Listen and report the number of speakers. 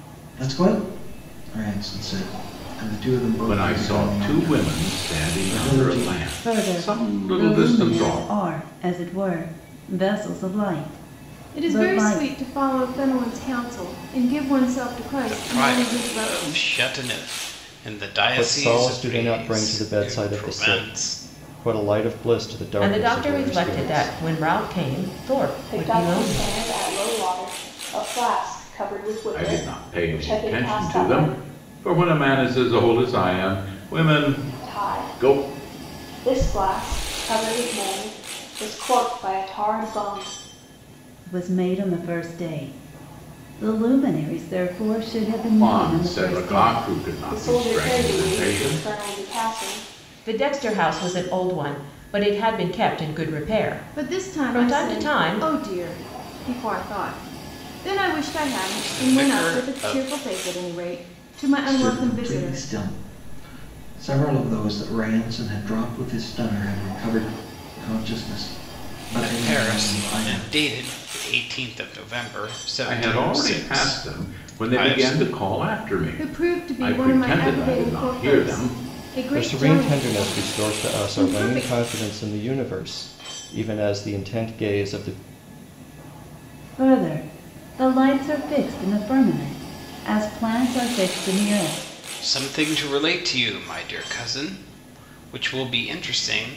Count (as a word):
eight